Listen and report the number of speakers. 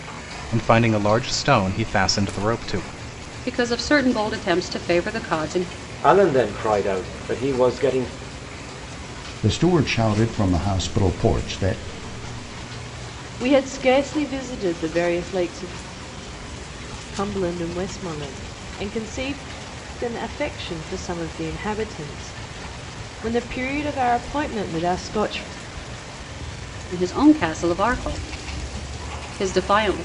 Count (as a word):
five